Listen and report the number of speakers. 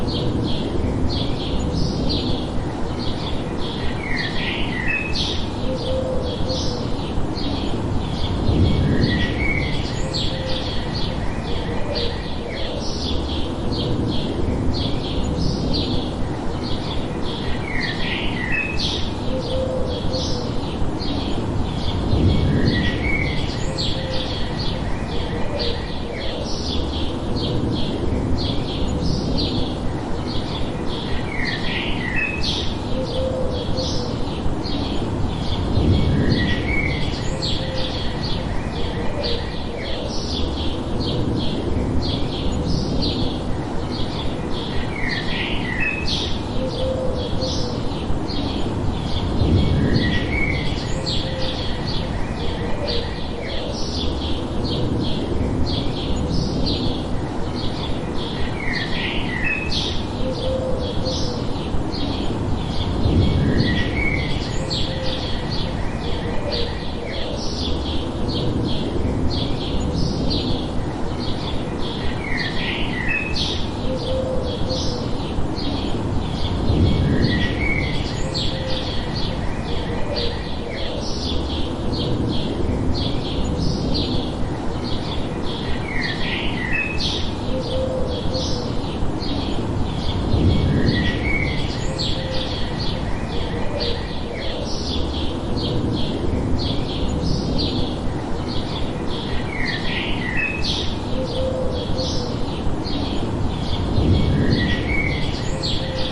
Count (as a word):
zero